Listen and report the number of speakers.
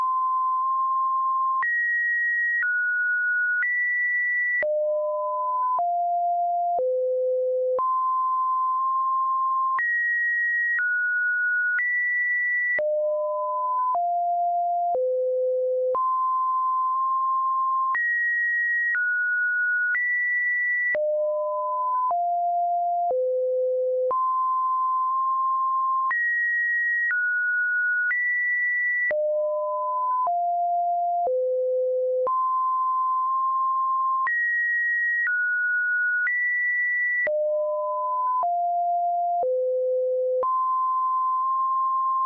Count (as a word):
zero